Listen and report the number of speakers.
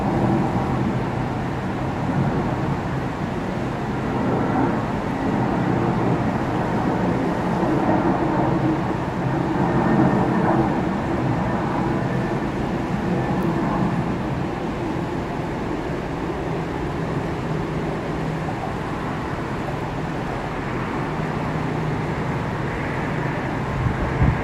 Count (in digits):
0